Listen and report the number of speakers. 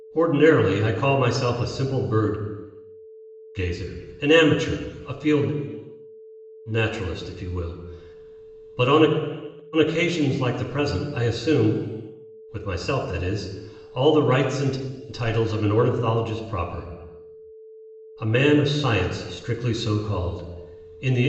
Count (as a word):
one